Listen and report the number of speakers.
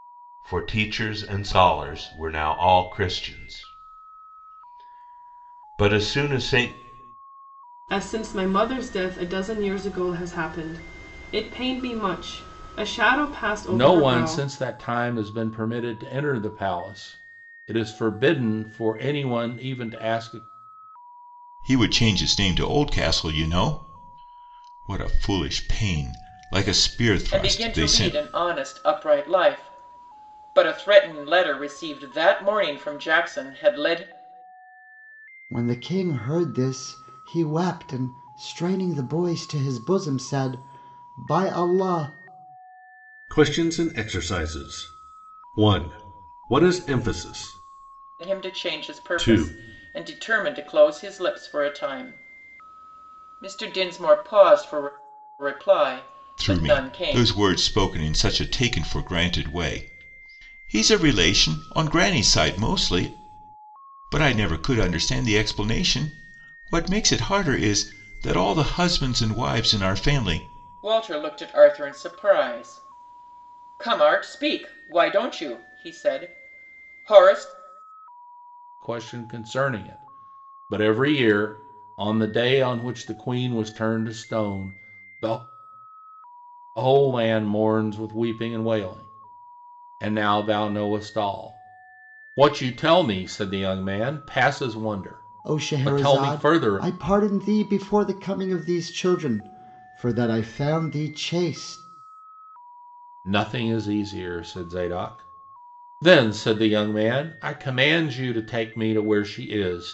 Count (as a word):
seven